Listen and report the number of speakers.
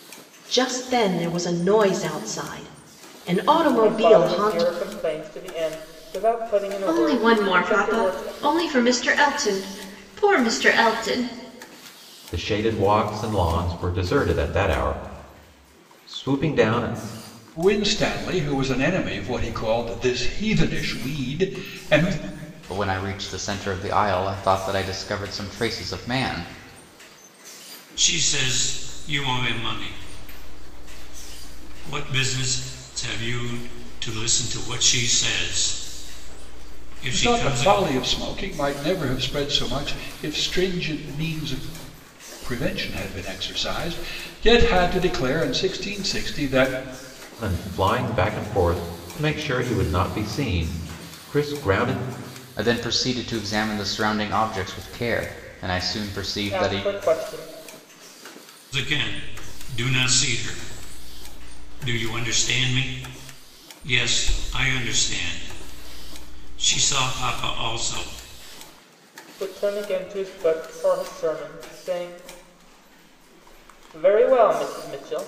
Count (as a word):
seven